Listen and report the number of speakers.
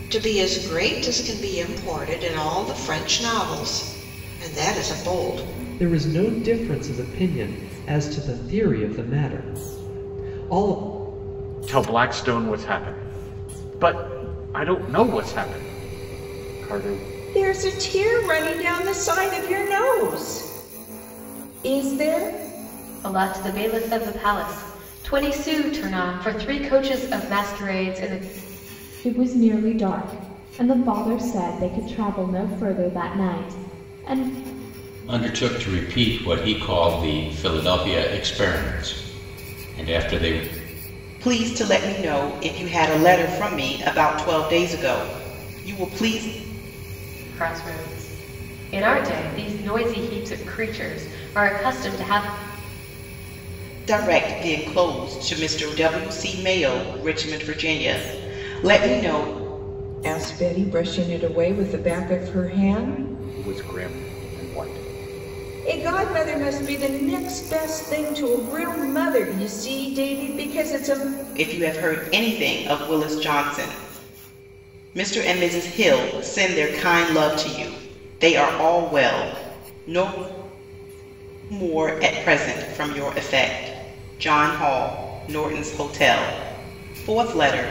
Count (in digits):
8